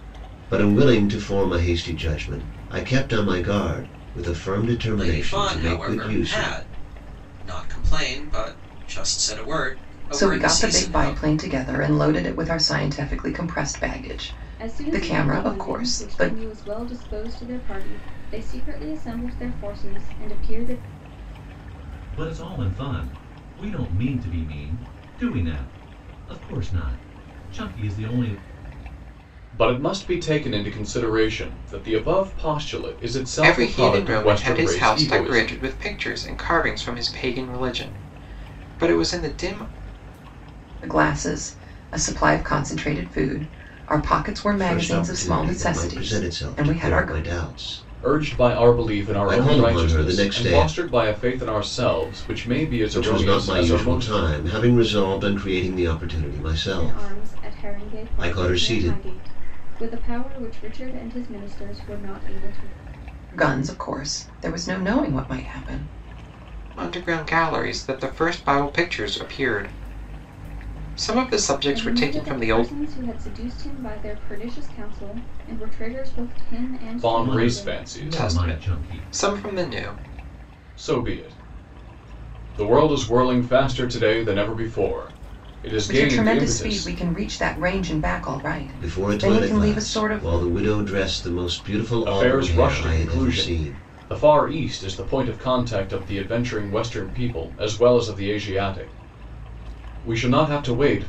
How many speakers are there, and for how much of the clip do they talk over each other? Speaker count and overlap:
7, about 23%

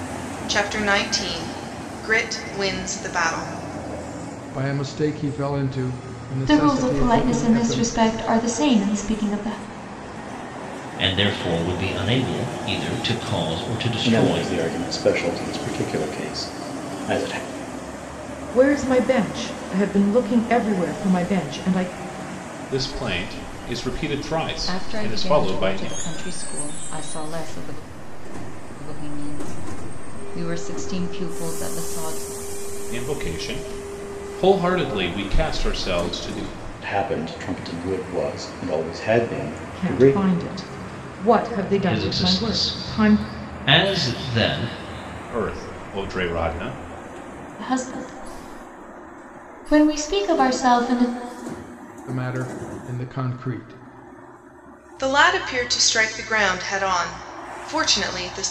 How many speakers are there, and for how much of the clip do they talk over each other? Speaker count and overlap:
8, about 9%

